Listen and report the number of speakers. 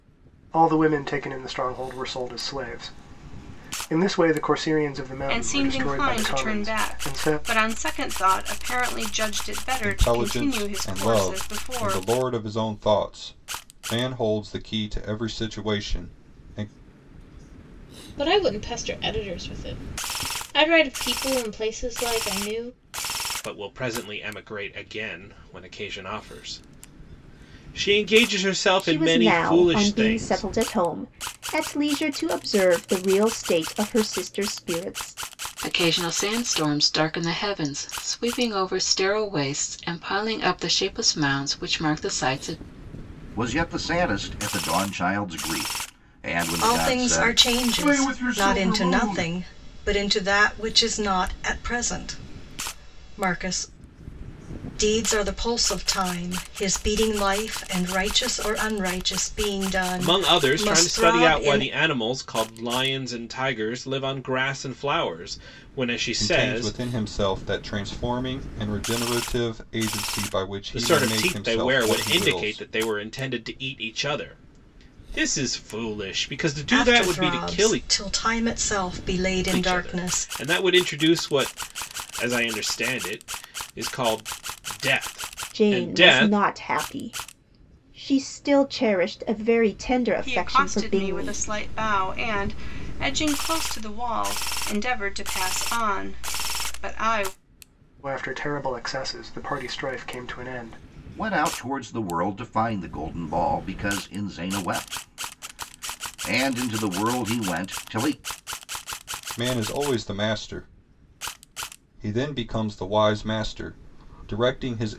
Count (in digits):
9